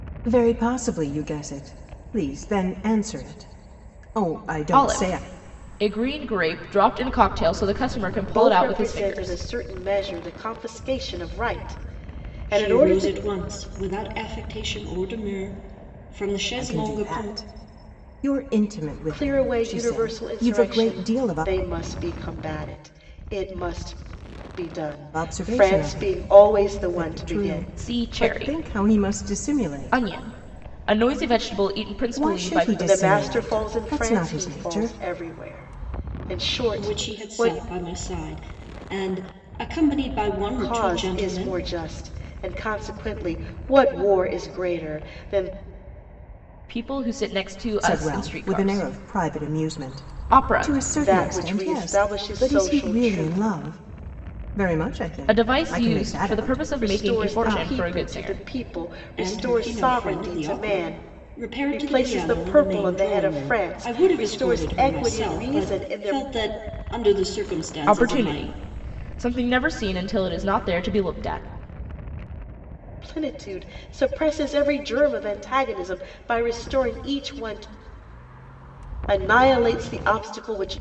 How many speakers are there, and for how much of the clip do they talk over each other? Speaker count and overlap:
four, about 38%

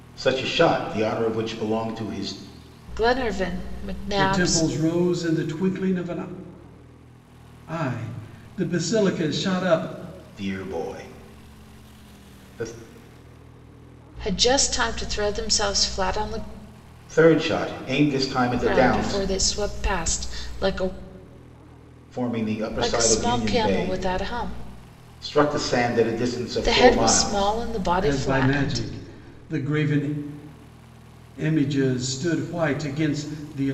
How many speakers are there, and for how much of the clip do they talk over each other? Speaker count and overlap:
three, about 13%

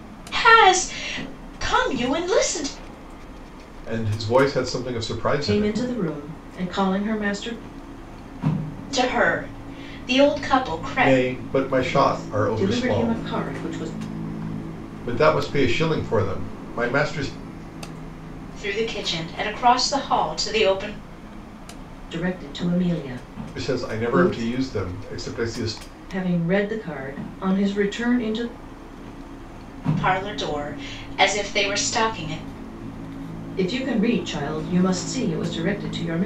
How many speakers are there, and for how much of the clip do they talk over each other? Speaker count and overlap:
three, about 9%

